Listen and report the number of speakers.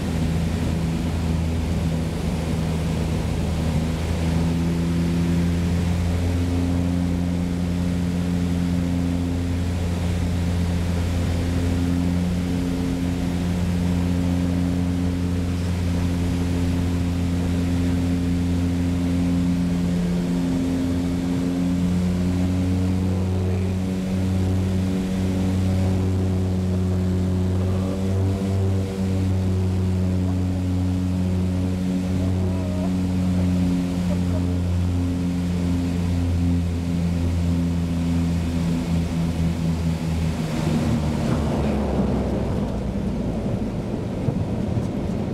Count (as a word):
zero